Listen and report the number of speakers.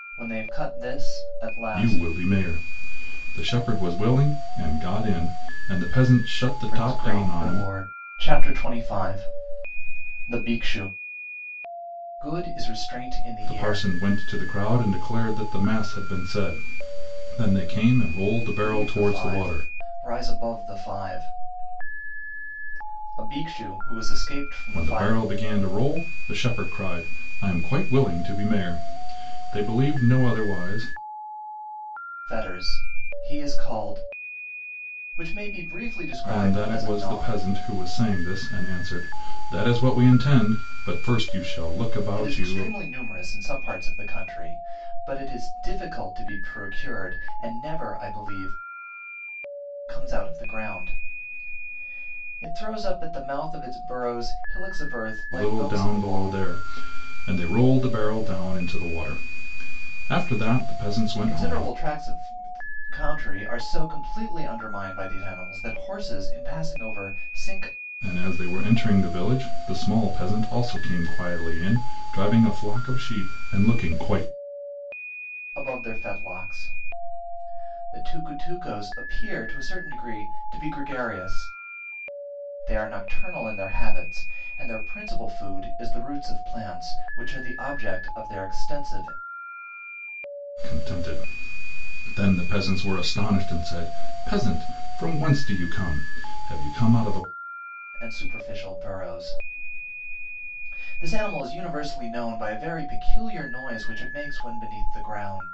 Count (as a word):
two